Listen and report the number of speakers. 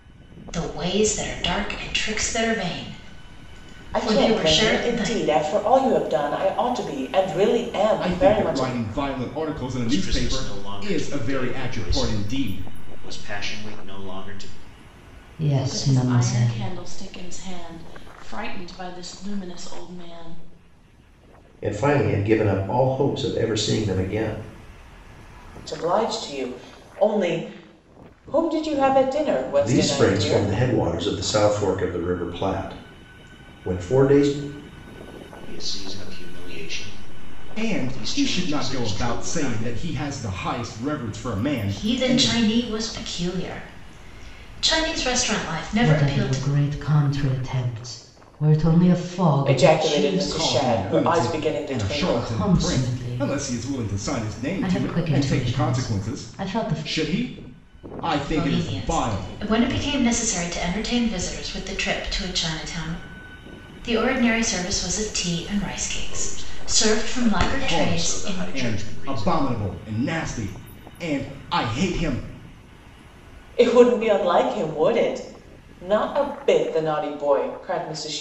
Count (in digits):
7